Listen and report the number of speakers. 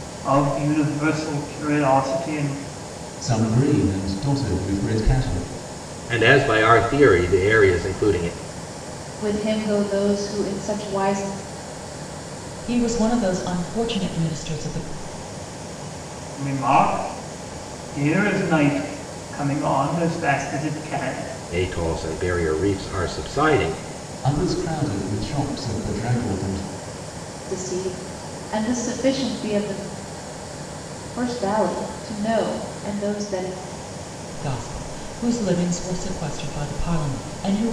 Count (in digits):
5